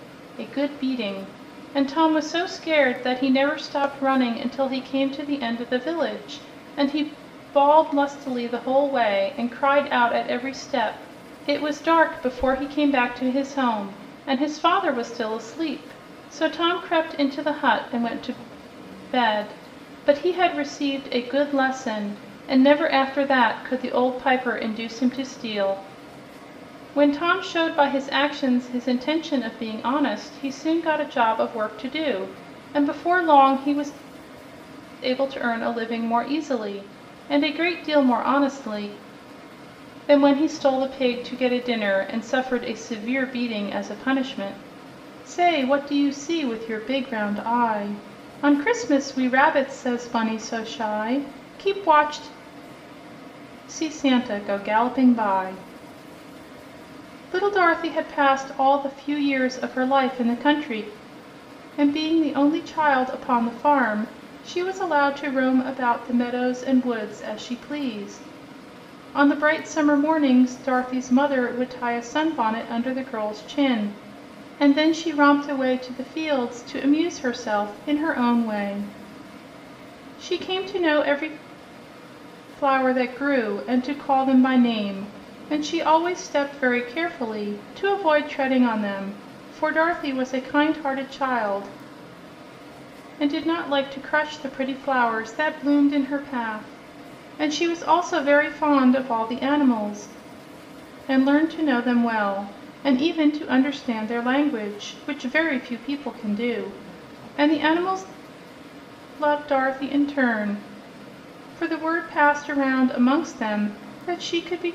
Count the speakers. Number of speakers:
one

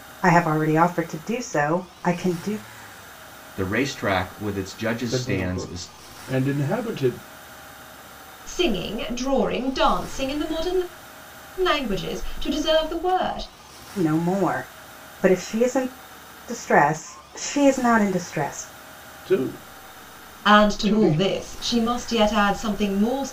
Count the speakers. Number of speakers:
four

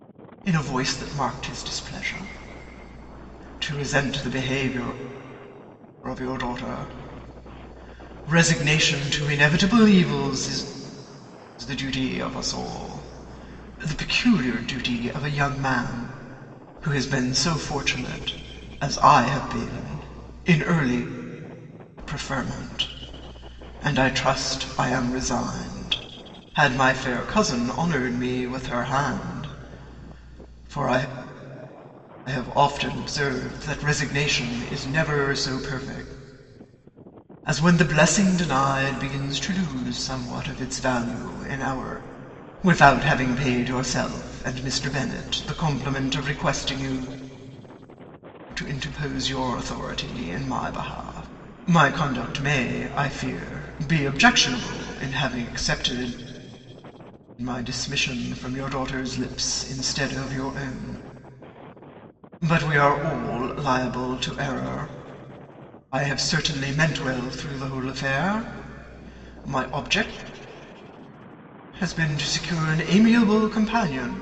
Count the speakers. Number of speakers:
one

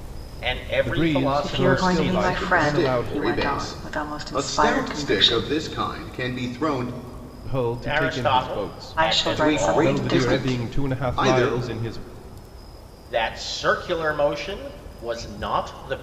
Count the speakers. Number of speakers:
four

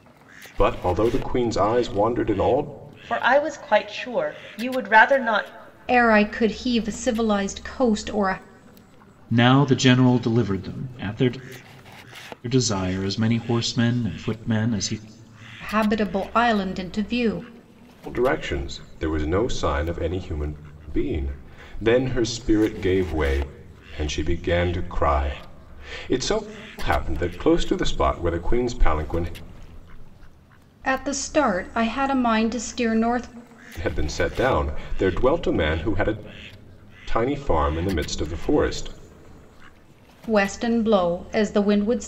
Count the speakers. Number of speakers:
four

